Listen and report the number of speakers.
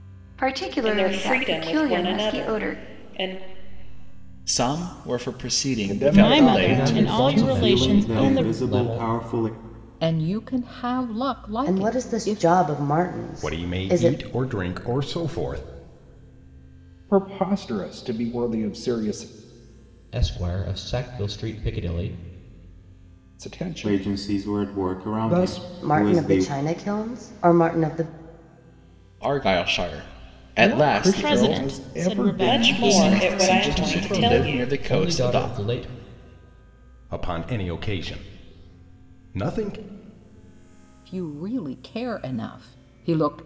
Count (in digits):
10